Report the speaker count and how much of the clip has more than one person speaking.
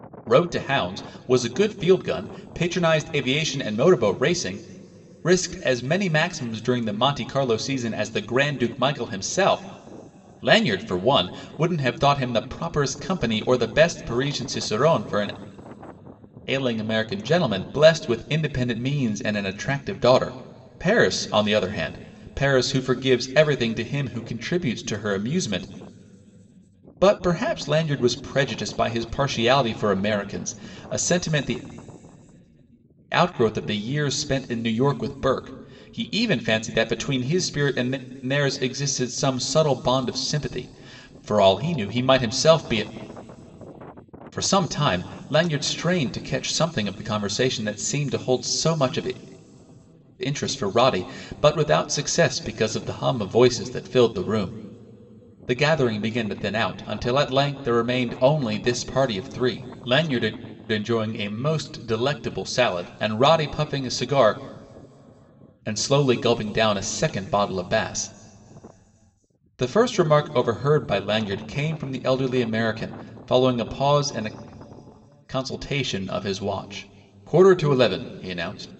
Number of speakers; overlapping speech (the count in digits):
1, no overlap